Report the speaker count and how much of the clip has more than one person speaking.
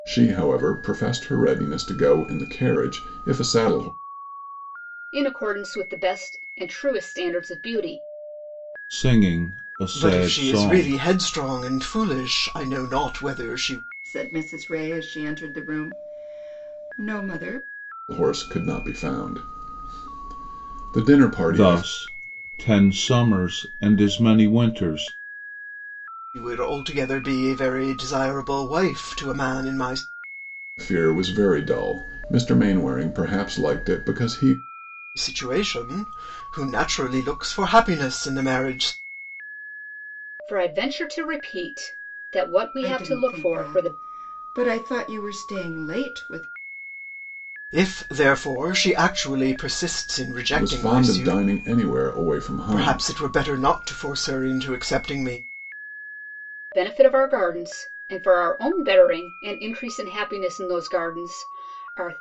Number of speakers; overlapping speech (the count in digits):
5, about 6%